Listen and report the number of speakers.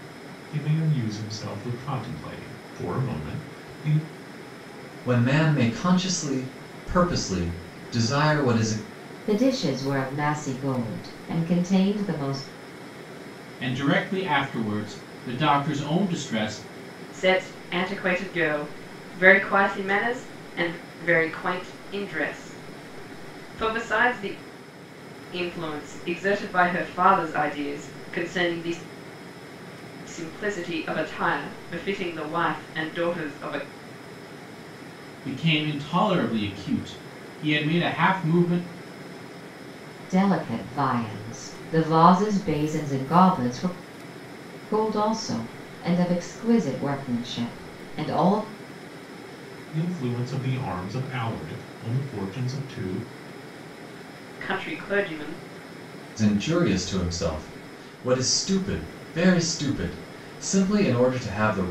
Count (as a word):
five